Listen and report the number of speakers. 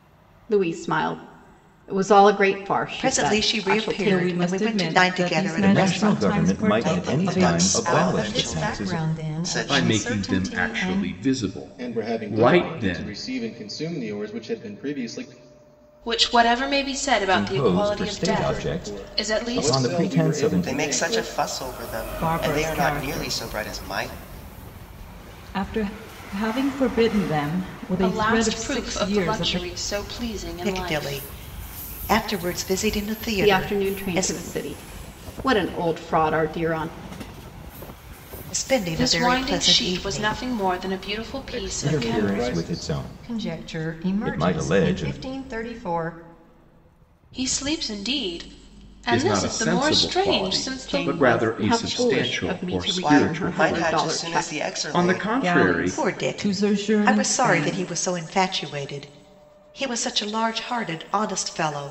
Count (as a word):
nine